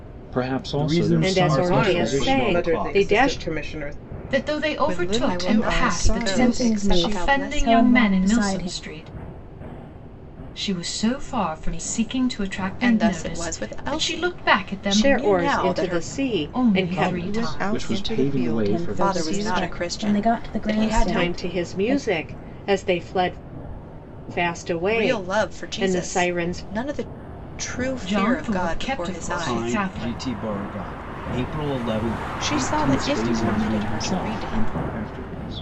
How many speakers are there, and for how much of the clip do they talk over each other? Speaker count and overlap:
8, about 65%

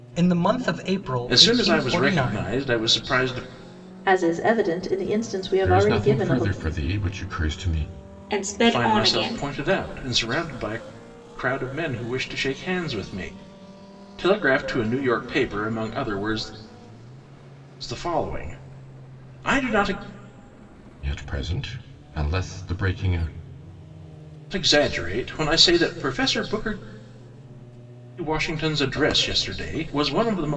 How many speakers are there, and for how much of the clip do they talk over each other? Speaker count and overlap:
5, about 10%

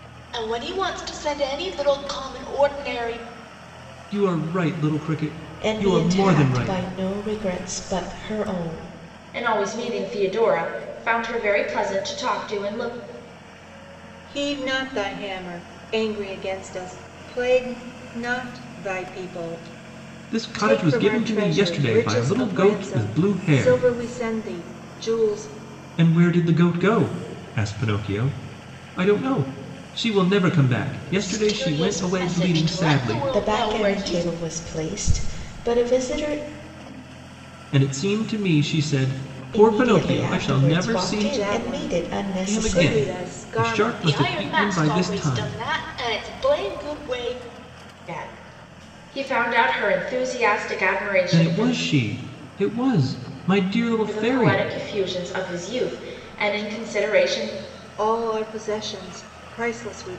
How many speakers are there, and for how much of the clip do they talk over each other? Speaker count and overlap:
5, about 25%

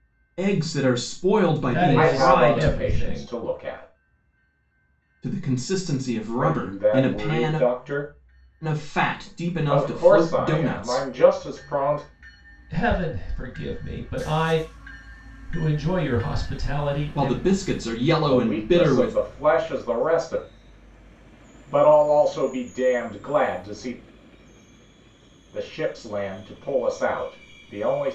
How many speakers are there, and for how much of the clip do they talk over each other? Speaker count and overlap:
3, about 20%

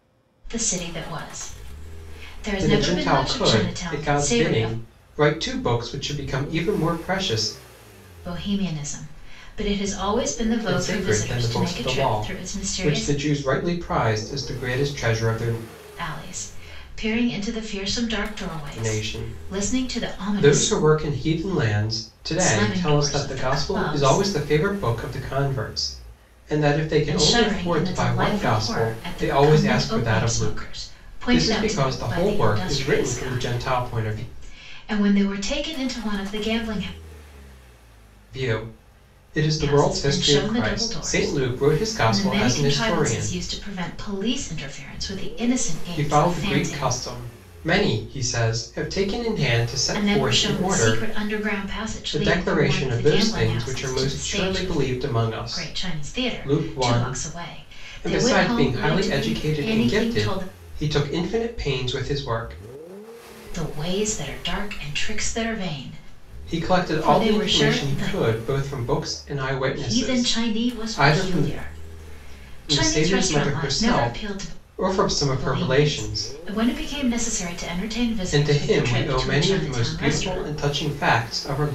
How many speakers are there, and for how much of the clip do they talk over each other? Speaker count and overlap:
2, about 45%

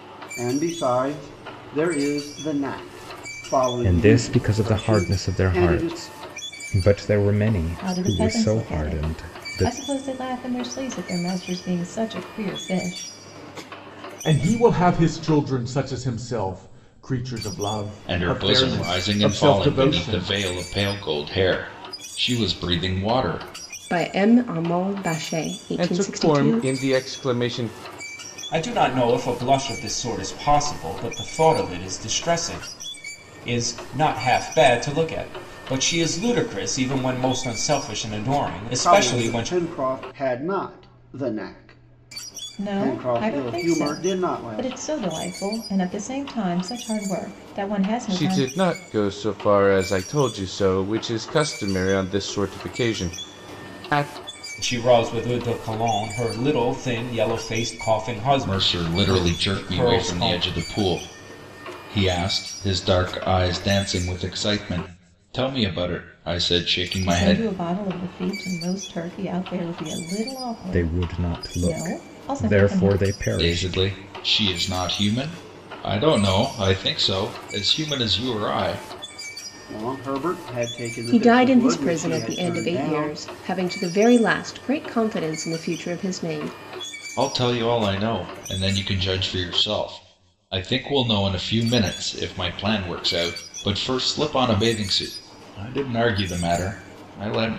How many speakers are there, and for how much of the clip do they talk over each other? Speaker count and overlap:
8, about 19%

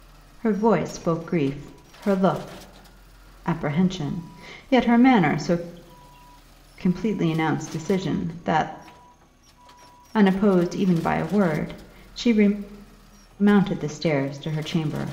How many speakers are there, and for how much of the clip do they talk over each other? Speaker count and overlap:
1, no overlap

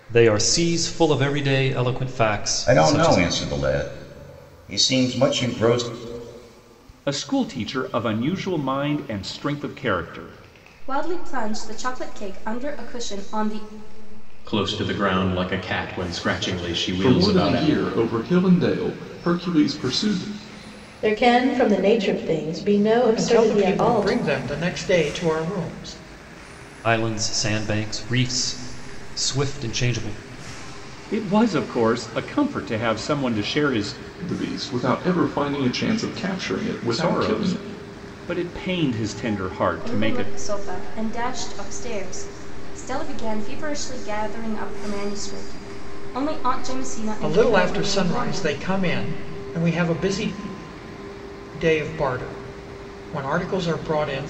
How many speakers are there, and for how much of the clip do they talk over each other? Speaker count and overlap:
8, about 9%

